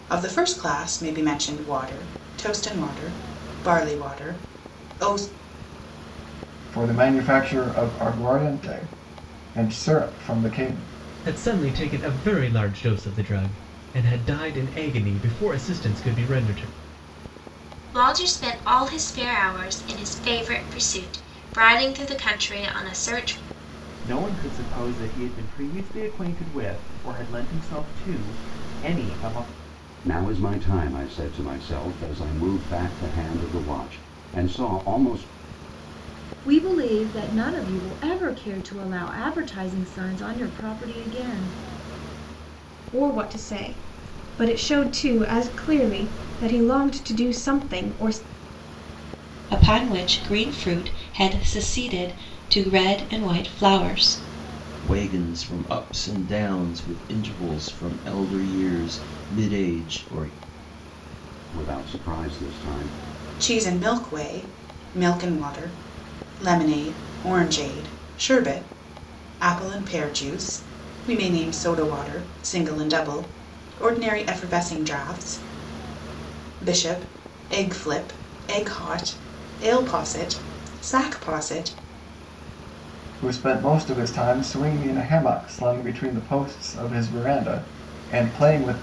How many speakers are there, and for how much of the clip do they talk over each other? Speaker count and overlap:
10, no overlap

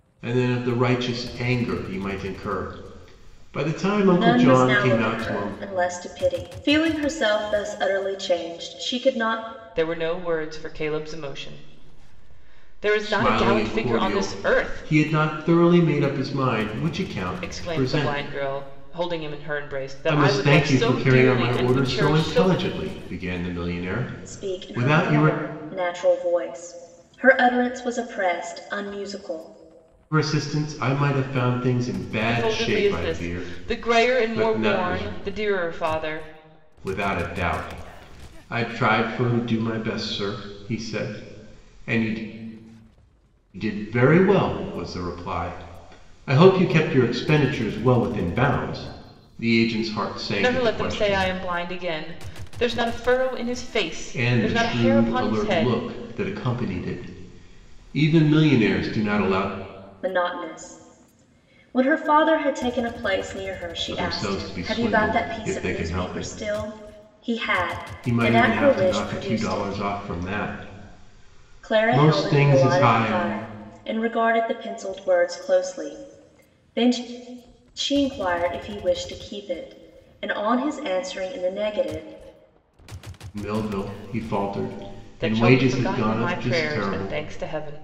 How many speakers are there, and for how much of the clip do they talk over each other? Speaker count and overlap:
3, about 24%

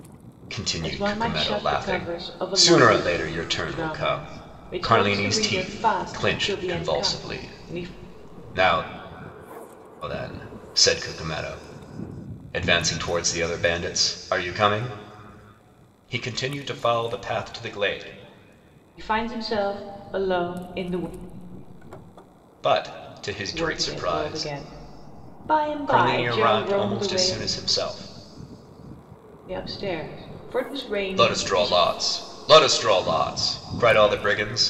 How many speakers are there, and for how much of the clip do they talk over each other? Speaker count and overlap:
2, about 26%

